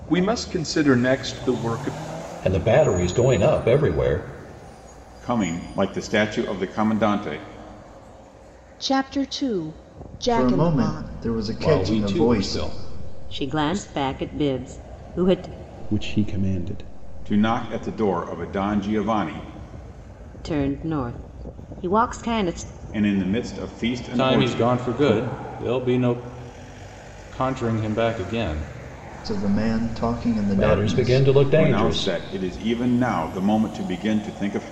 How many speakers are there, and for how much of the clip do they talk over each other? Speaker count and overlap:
8, about 15%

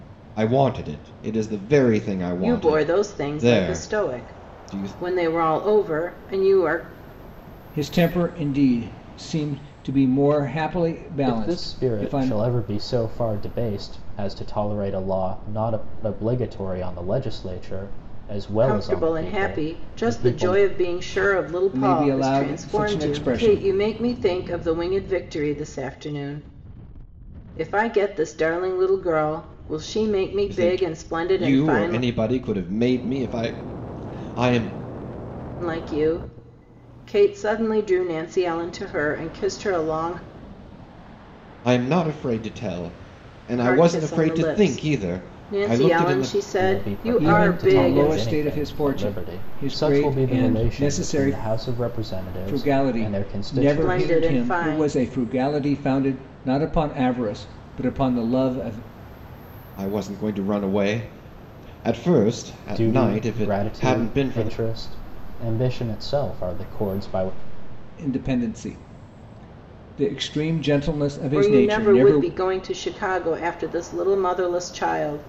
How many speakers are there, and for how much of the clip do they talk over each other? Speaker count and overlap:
4, about 29%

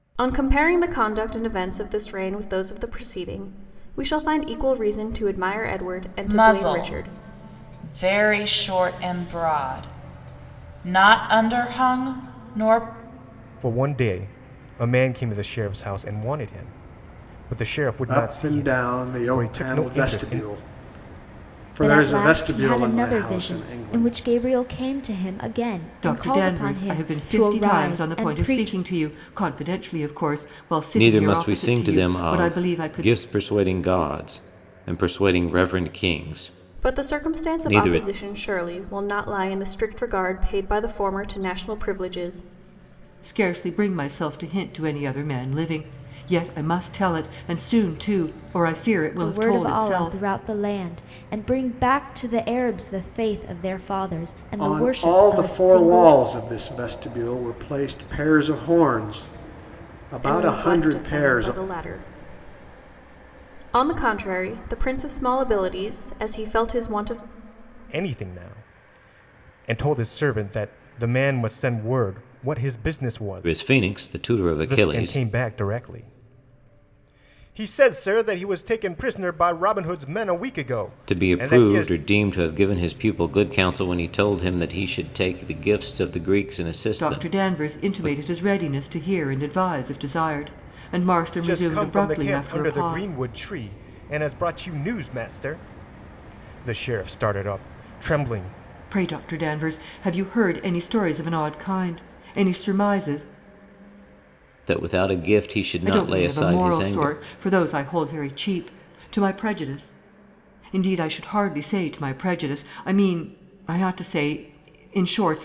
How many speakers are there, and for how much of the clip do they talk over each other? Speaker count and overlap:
7, about 20%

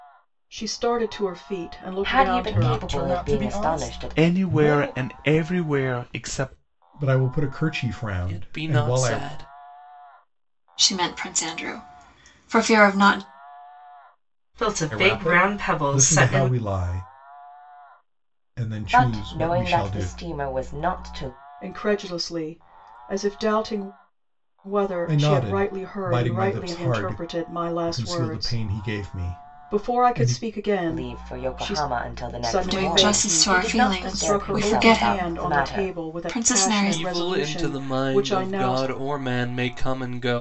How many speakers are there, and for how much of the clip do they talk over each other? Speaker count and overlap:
8, about 44%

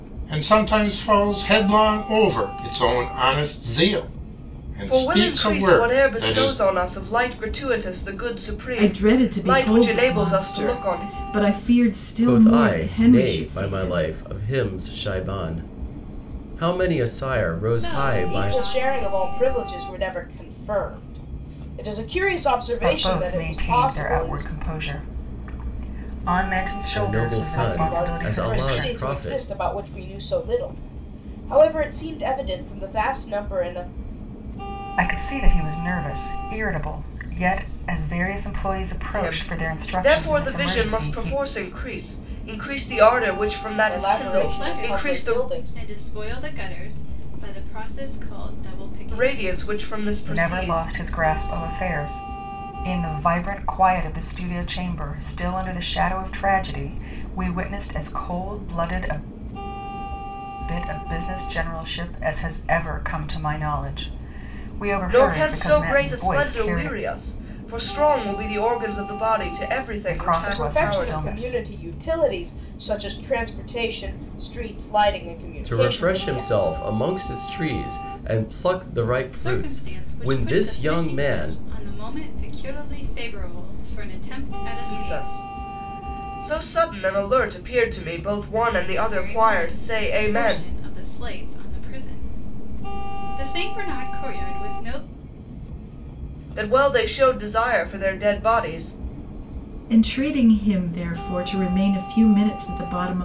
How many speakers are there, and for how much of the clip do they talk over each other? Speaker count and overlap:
7, about 26%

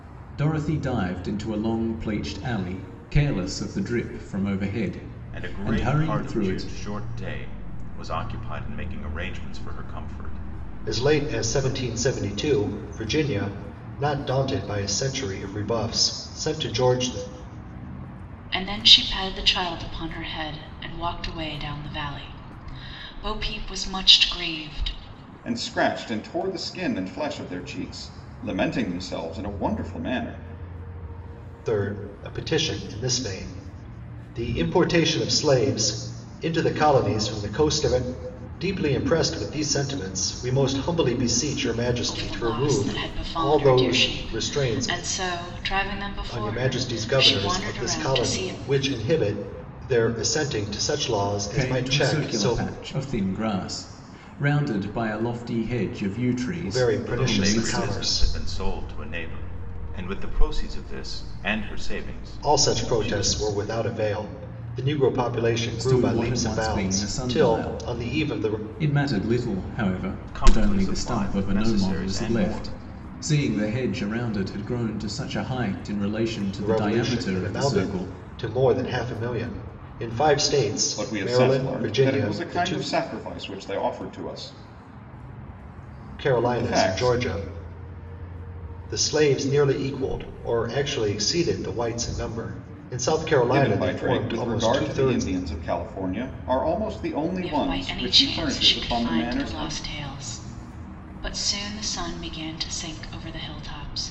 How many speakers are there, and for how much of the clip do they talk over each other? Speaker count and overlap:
5, about 24%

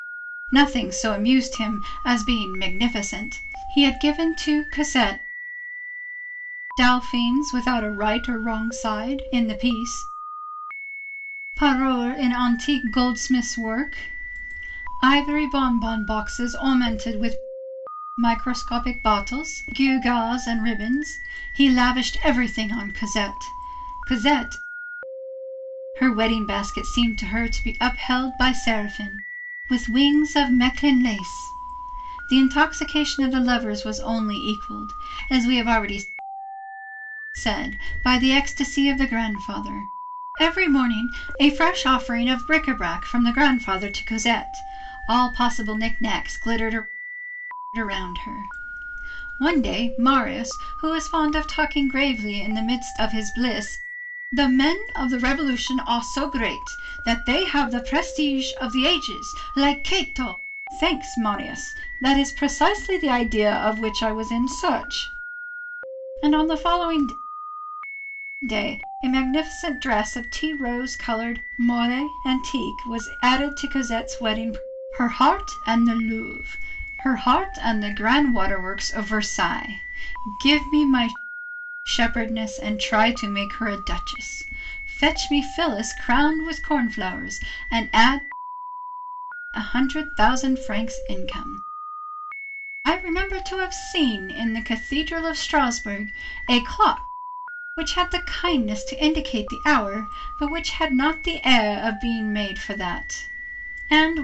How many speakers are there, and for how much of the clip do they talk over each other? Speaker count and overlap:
1, no overlap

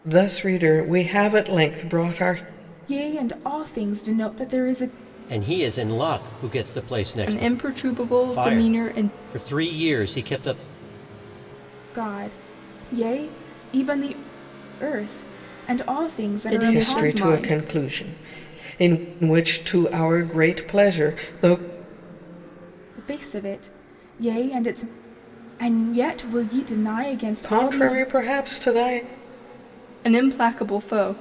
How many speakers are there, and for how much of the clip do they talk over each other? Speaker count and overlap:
4, about 10%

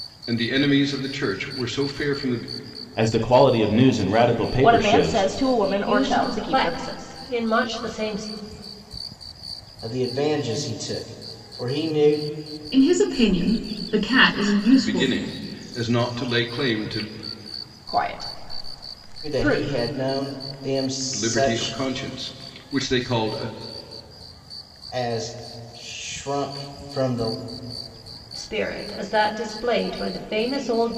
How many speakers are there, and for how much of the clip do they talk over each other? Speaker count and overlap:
6, about 10%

